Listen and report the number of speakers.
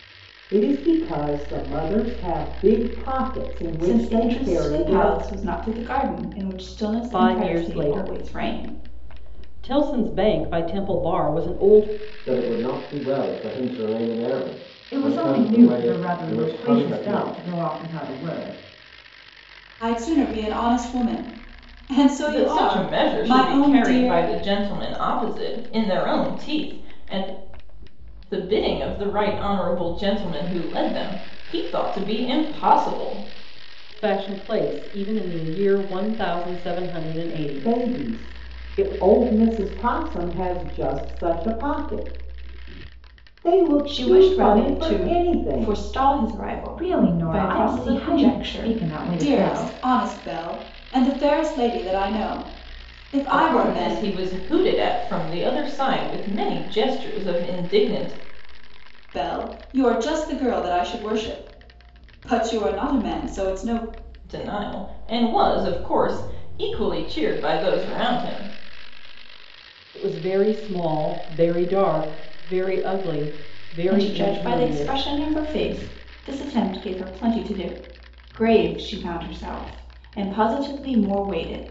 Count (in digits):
7